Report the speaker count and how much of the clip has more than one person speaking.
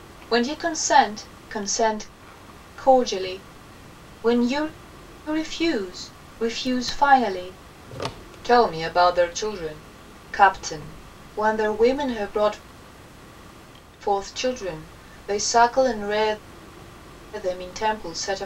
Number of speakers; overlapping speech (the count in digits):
1, no overlap